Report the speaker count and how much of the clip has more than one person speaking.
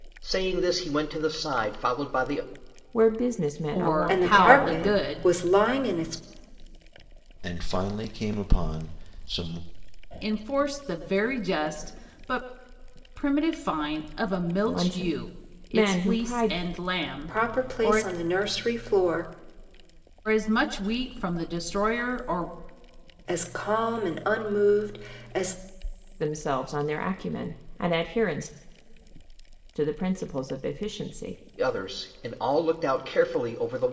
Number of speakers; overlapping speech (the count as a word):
five, about 12%